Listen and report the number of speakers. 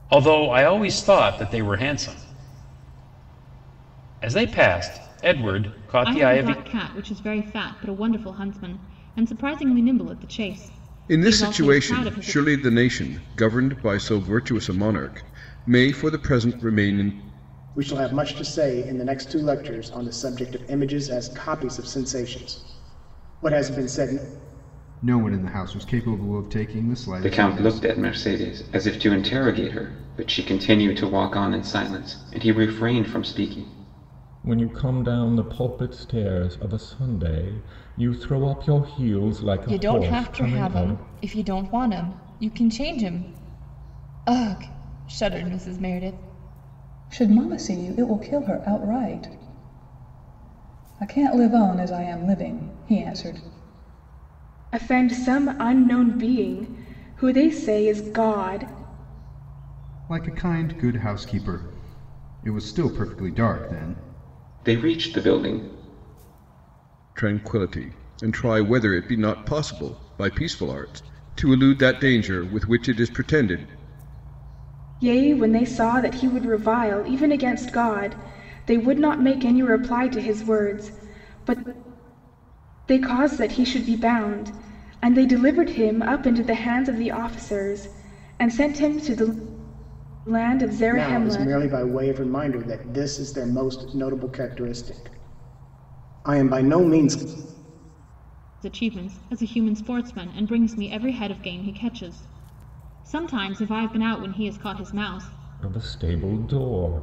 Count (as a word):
ten